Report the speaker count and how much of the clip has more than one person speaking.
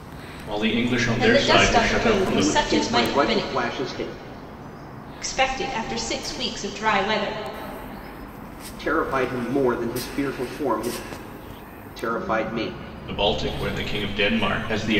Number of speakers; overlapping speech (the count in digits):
3, about 16%